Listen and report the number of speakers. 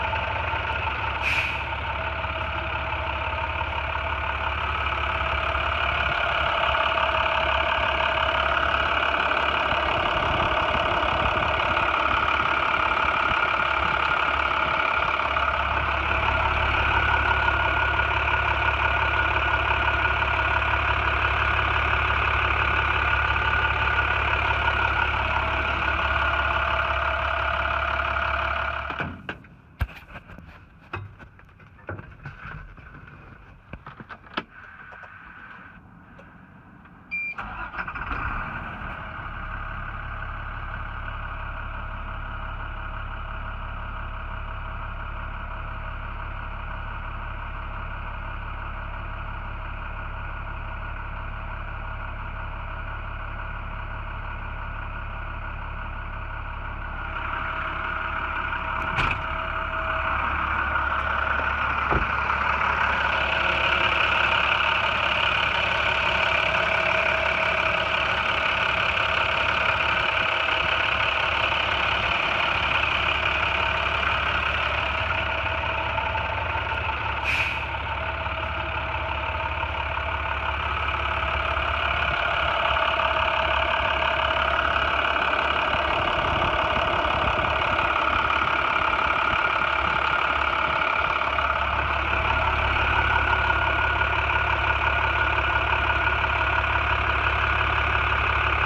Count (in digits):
0